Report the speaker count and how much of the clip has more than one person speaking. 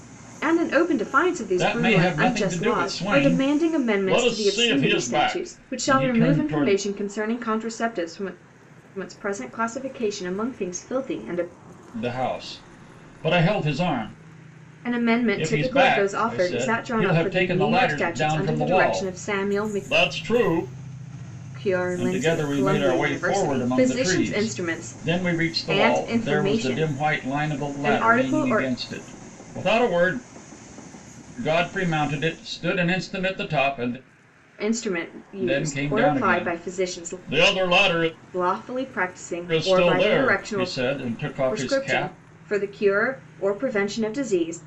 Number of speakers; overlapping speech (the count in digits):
2, about 43%